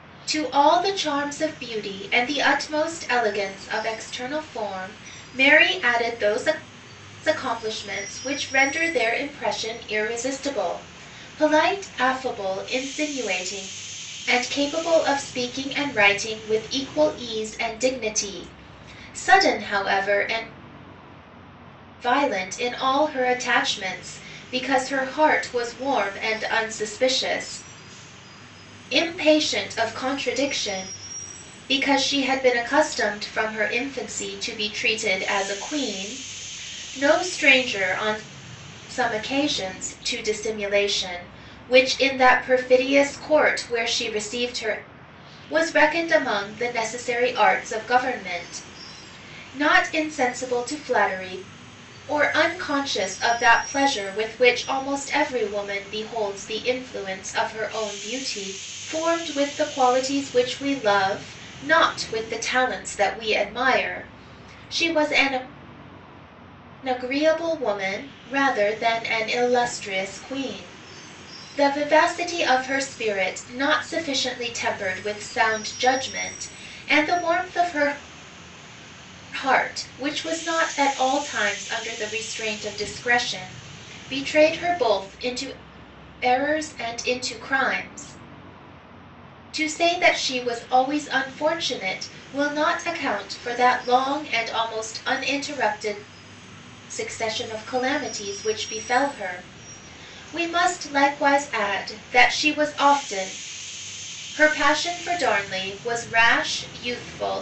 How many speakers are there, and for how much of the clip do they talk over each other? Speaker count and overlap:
one, no overlap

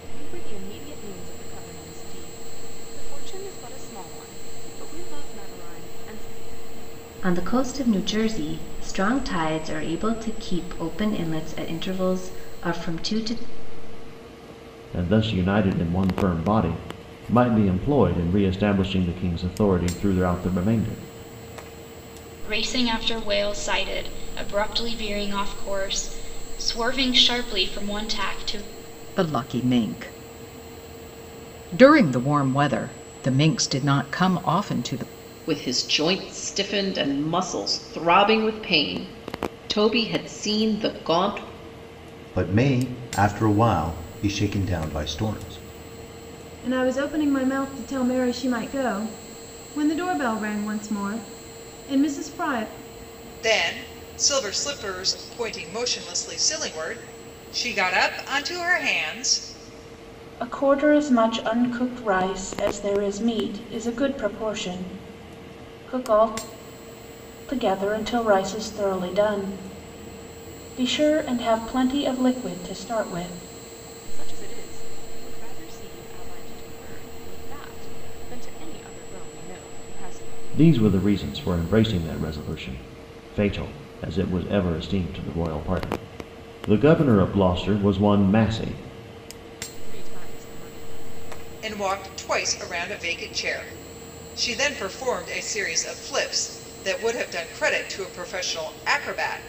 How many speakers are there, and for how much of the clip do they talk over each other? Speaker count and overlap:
ten, no overlap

